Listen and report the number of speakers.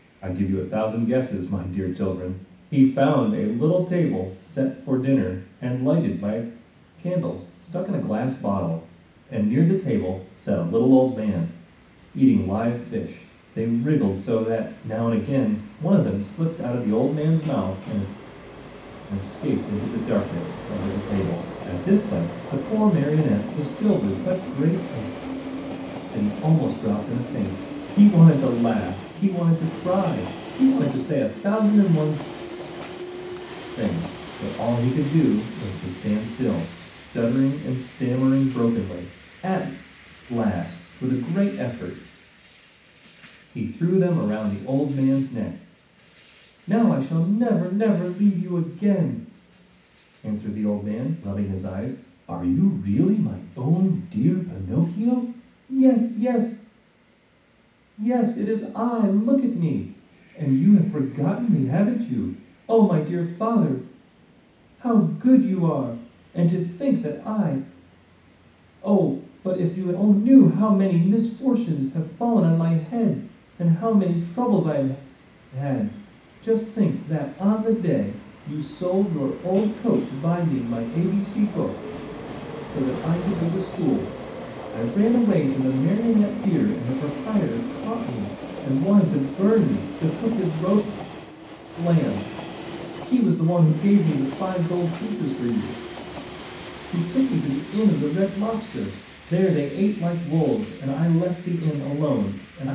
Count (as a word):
one